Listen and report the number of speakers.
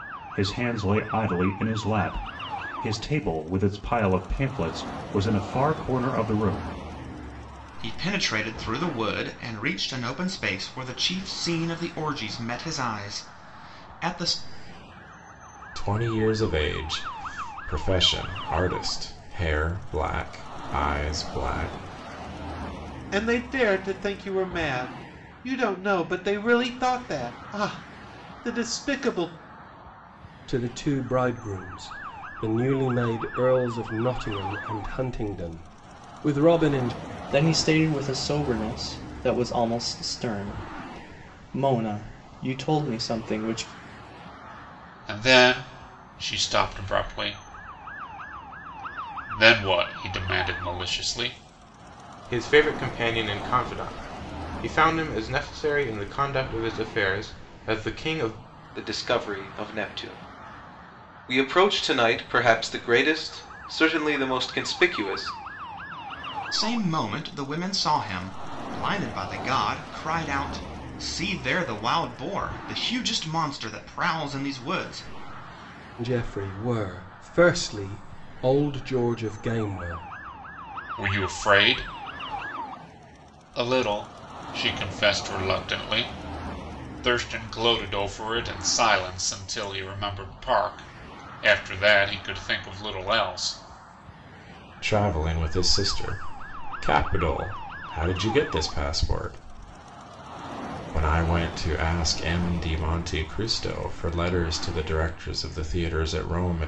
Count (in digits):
9